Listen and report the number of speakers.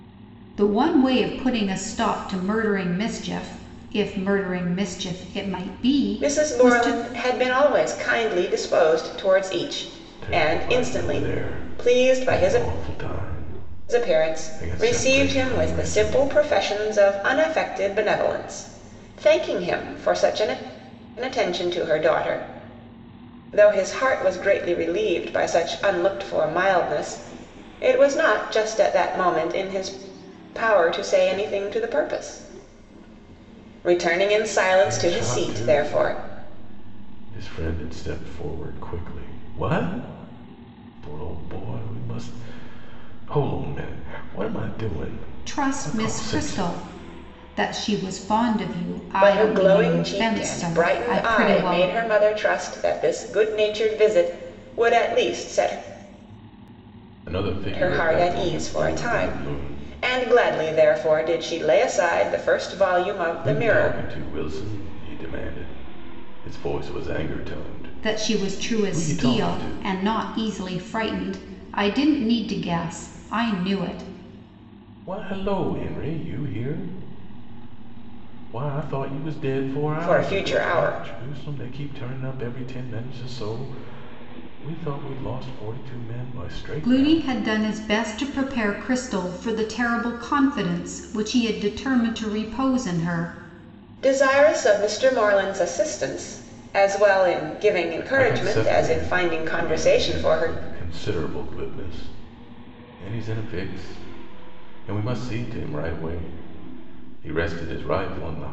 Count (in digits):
3